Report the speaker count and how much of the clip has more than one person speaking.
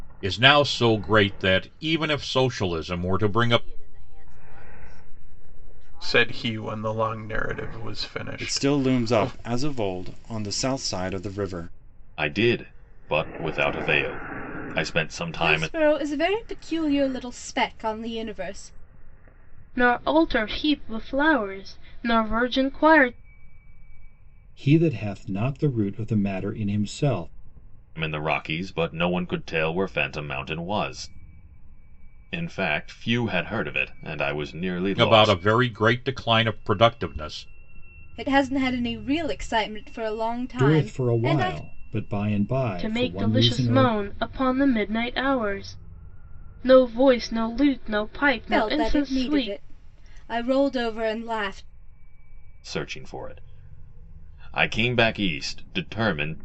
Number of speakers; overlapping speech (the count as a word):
eight, about 11%